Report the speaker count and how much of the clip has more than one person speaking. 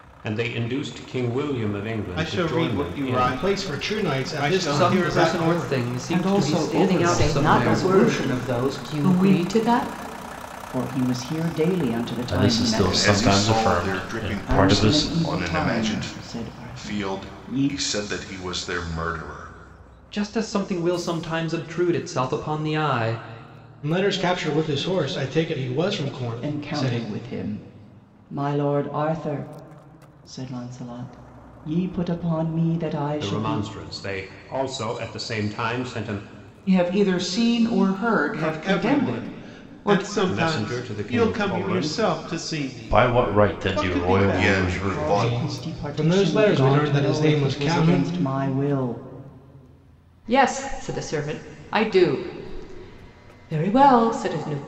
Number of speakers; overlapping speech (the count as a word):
nine, about 40%